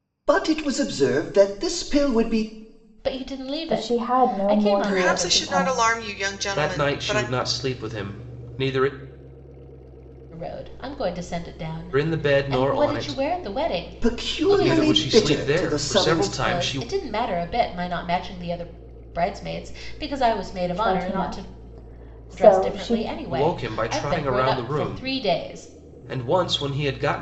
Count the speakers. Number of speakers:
five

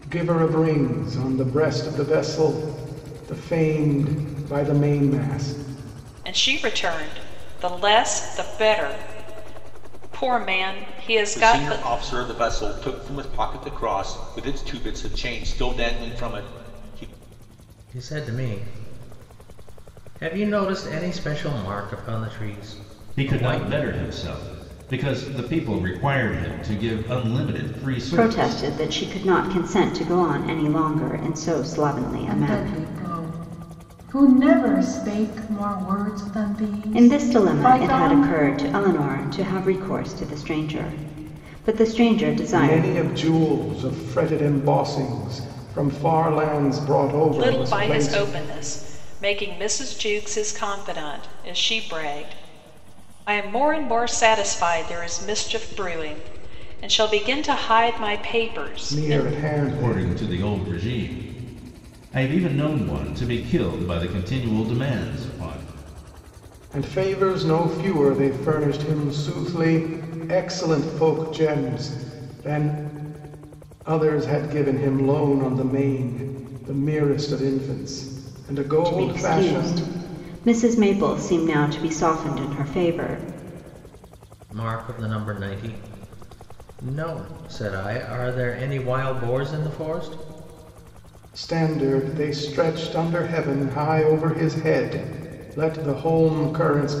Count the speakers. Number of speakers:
seven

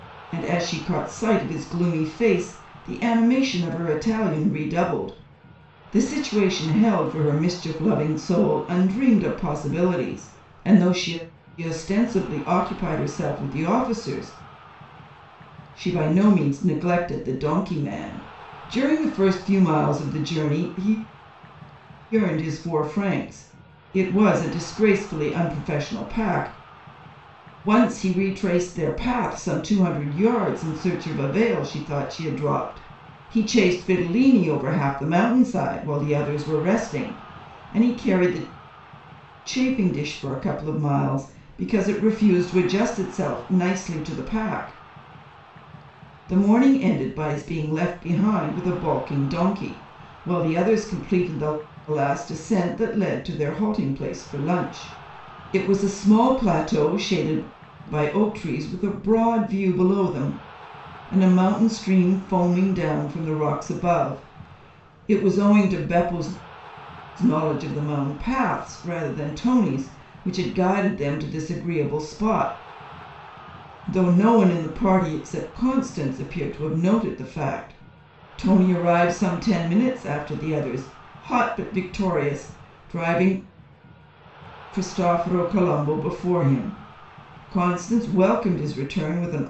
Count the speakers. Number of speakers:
one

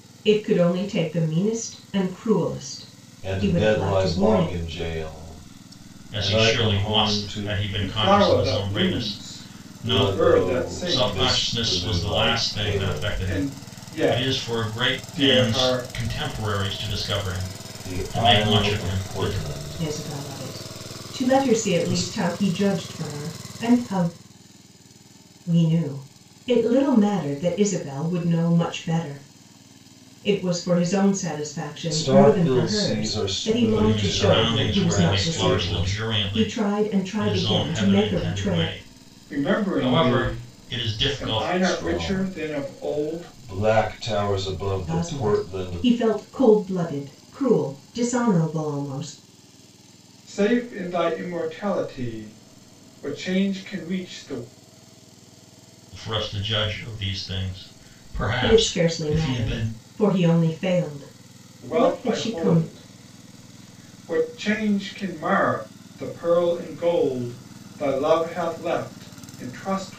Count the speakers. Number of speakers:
four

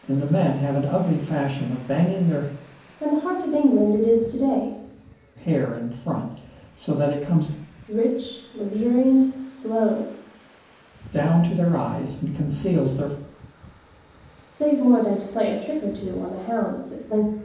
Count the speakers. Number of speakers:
two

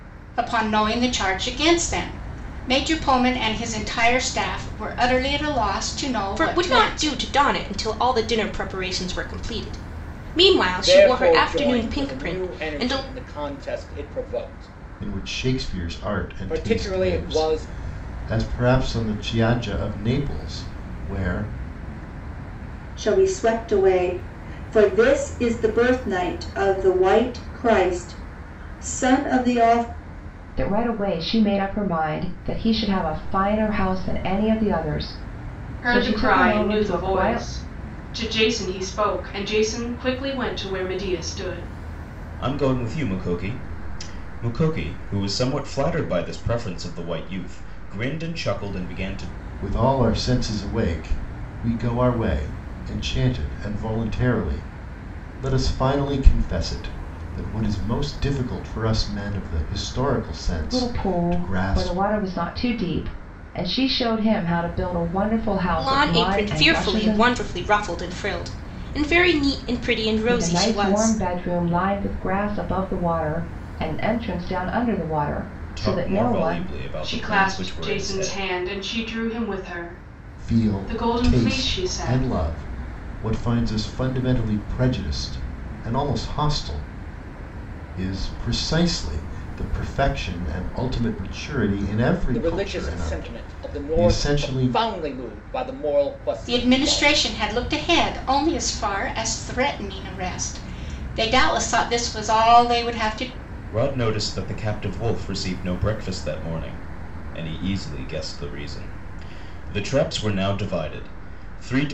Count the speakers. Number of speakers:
eight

